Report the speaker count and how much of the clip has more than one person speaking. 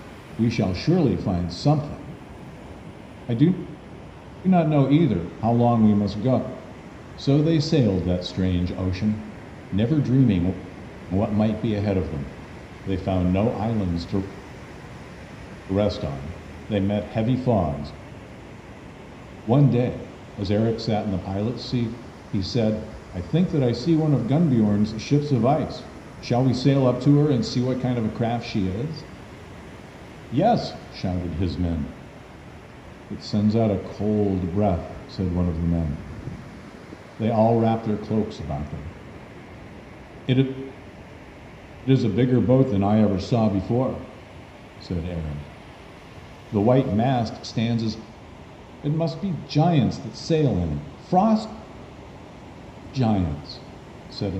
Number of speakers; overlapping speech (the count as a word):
one, no overlap